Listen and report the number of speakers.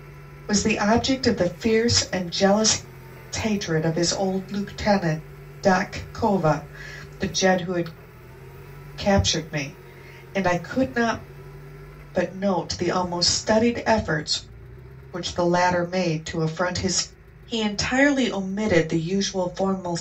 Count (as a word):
one